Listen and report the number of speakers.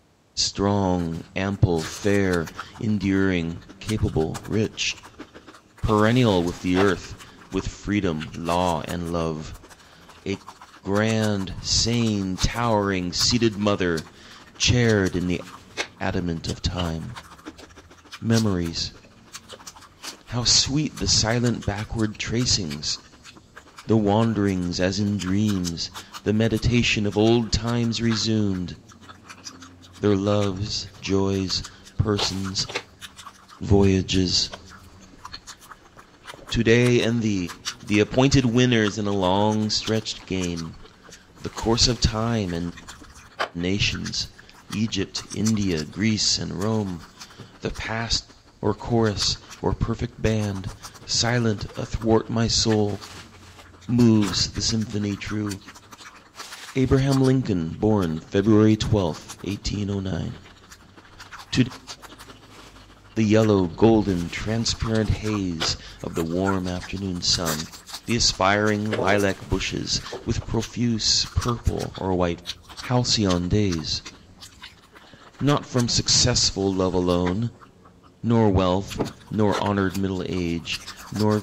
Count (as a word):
one